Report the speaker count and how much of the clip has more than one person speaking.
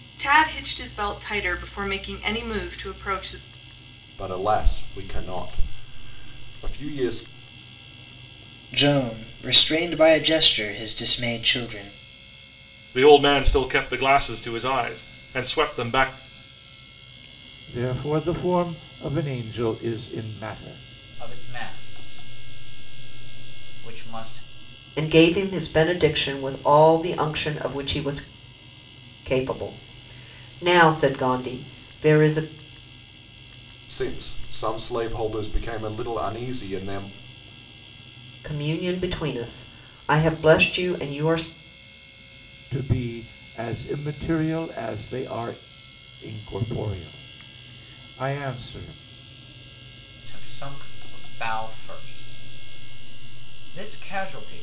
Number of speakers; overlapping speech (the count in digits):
7, no overlap